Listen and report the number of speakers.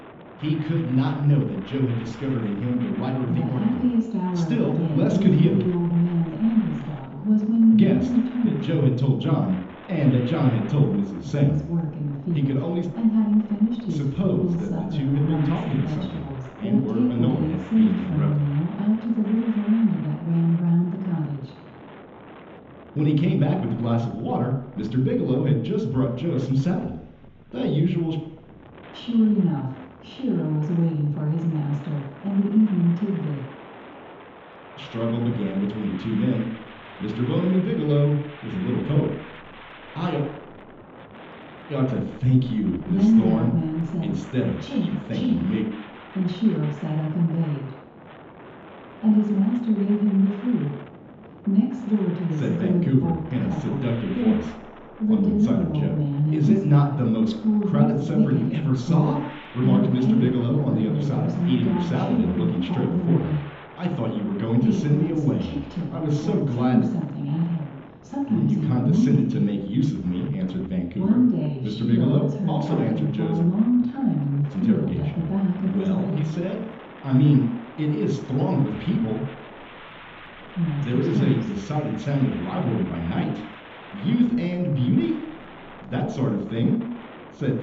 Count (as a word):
two